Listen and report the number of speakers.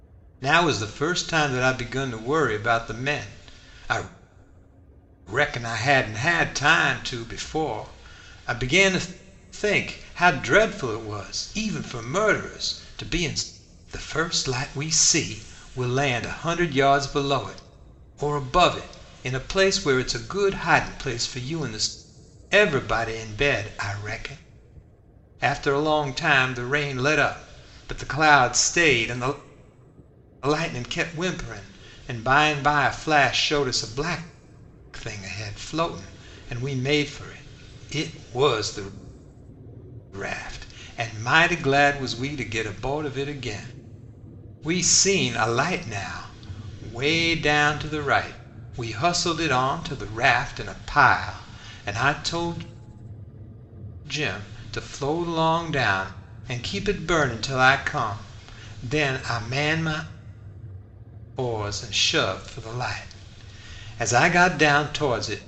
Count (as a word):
one